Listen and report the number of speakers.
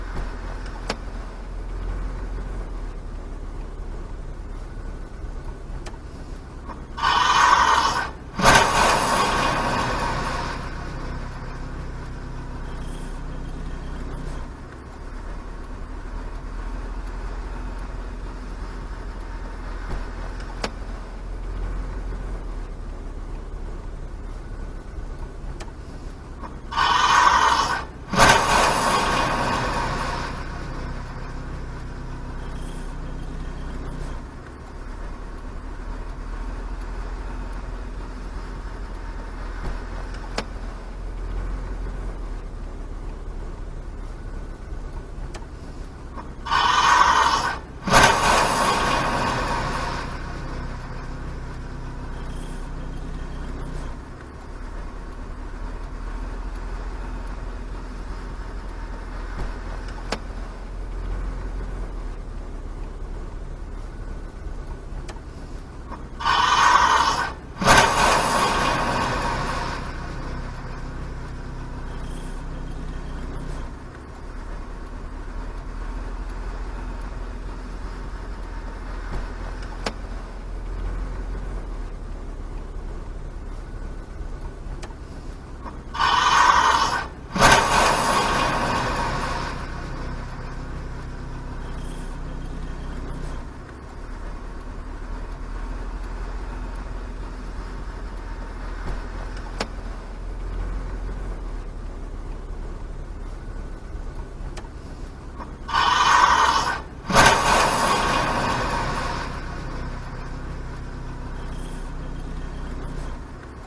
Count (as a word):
zero